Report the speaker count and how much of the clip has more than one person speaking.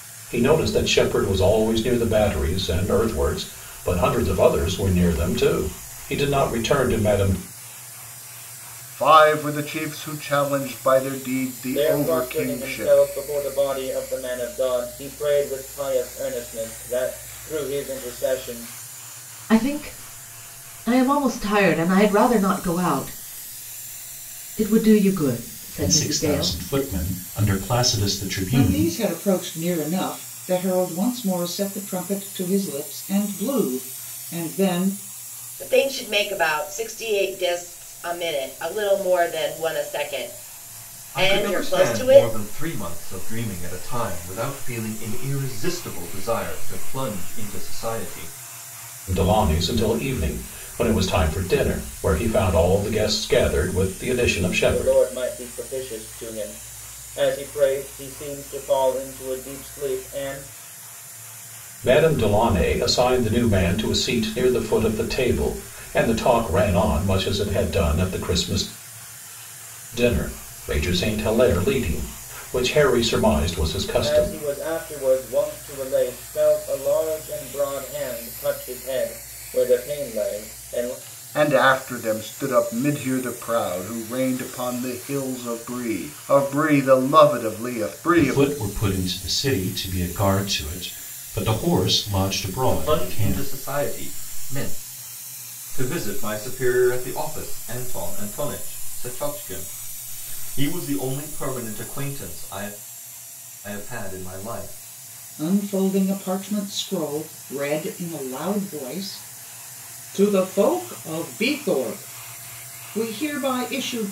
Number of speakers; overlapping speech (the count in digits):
8, about 5%